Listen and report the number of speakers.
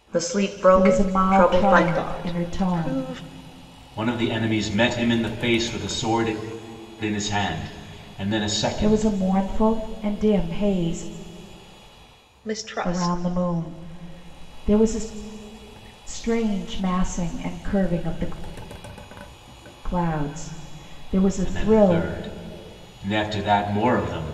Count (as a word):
four